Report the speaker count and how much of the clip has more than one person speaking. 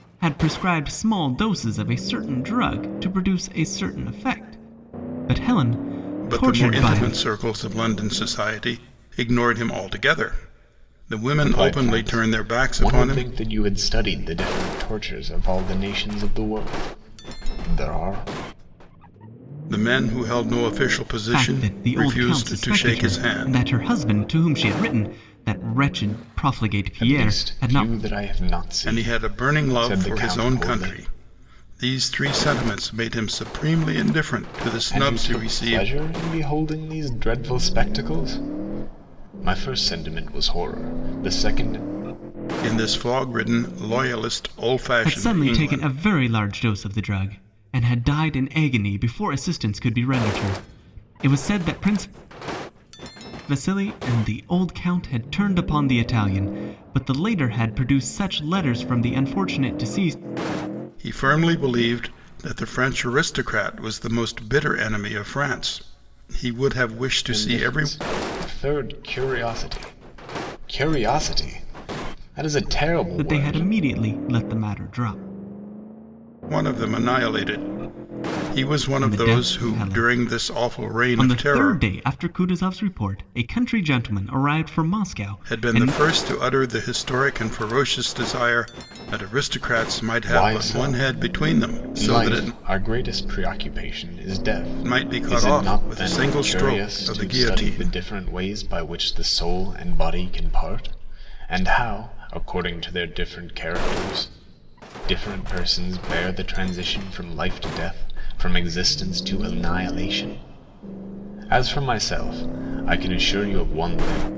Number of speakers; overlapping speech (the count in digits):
3, about 18%